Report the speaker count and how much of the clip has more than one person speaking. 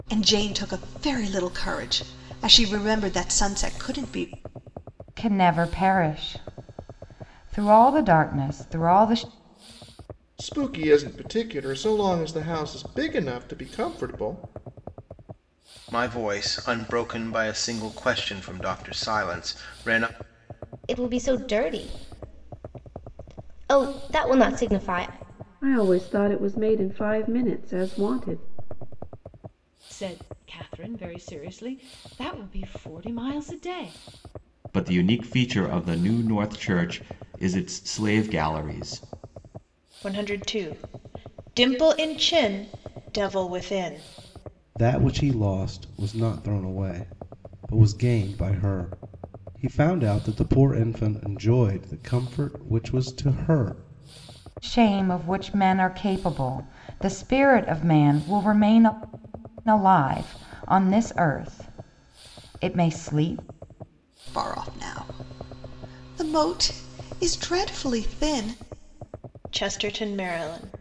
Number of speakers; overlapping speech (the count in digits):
10, no overlap